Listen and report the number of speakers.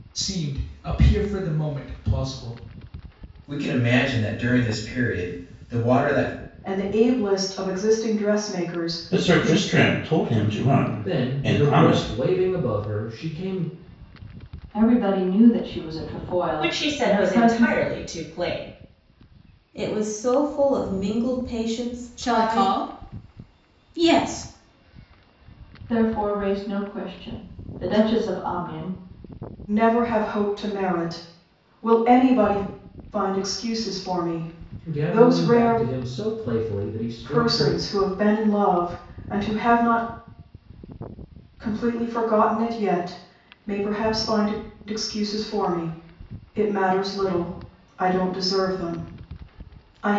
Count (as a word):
nine